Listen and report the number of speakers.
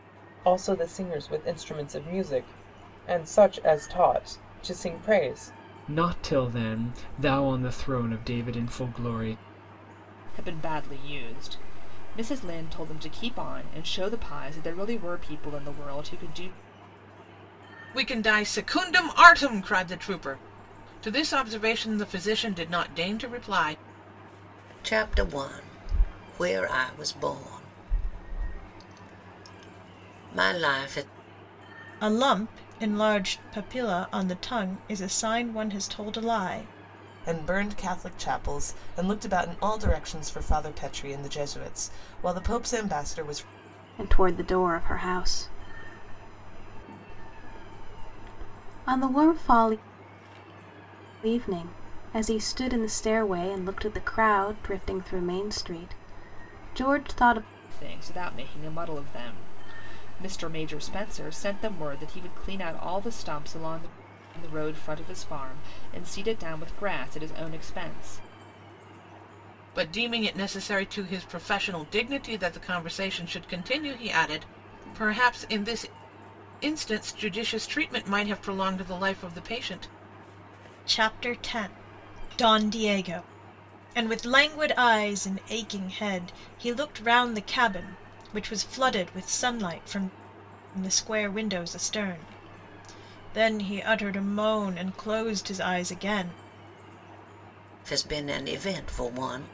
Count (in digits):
8